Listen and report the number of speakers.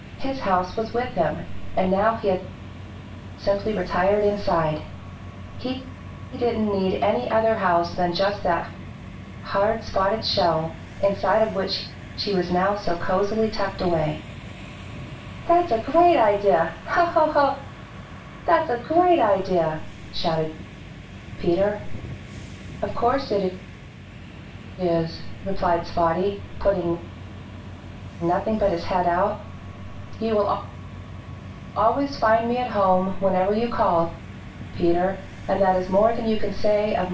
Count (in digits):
1